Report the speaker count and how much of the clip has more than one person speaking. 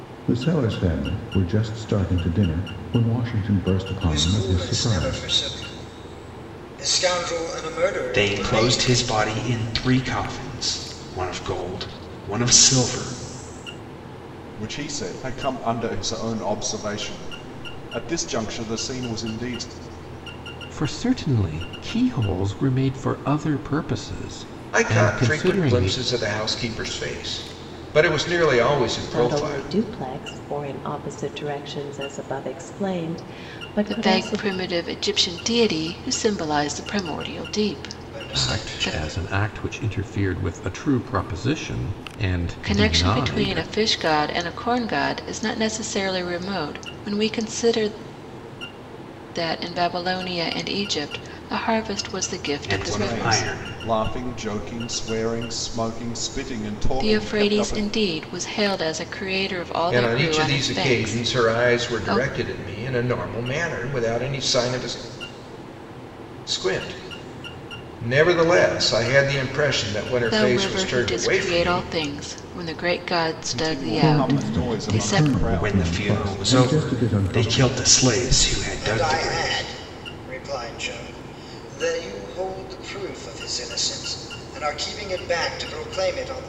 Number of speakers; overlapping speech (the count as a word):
eight, about 21%